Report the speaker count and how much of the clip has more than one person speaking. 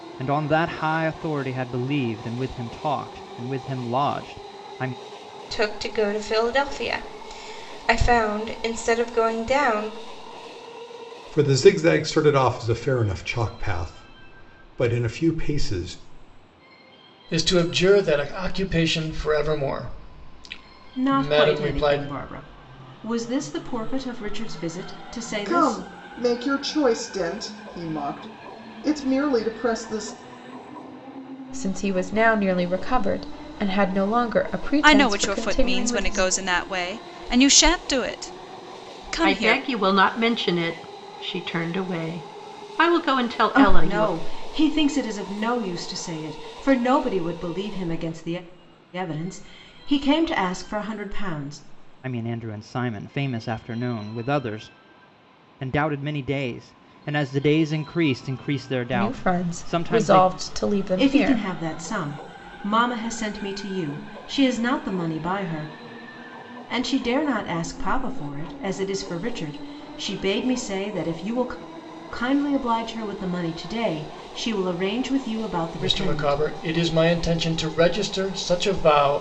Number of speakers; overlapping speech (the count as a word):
nine, about 8%